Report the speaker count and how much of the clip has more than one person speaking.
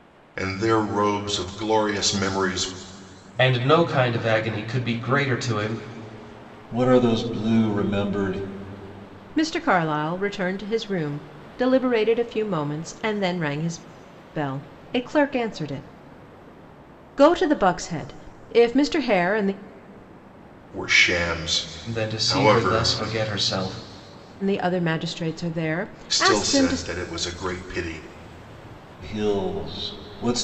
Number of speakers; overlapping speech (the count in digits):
4, about 7%